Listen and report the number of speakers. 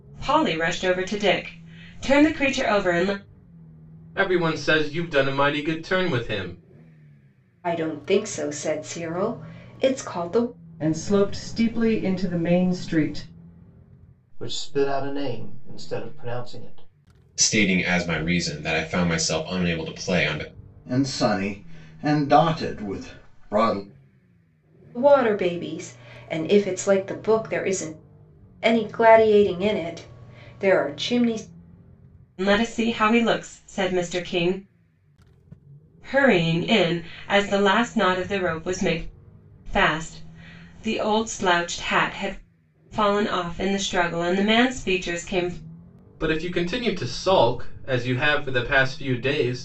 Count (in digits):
7